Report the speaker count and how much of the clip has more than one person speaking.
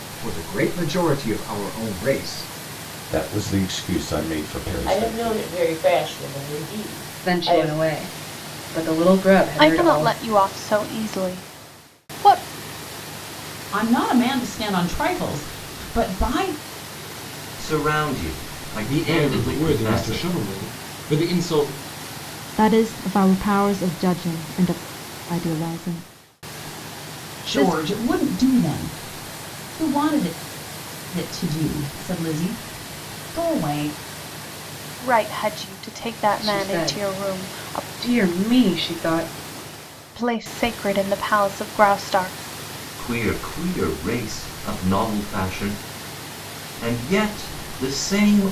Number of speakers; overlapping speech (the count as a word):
nine, about 11%